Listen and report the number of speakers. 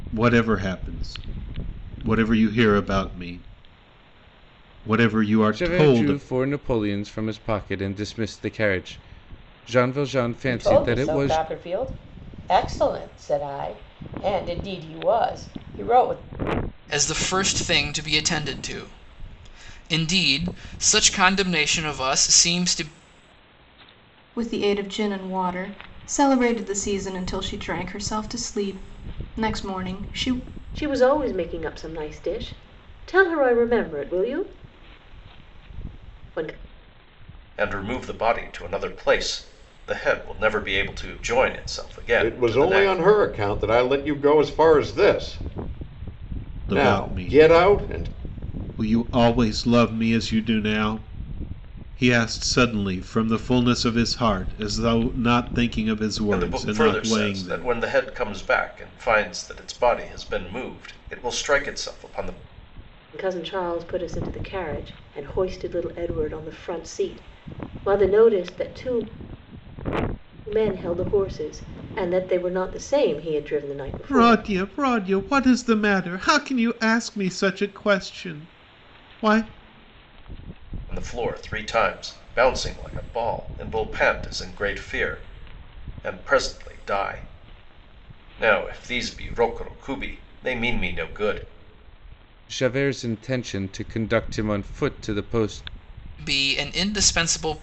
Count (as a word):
eight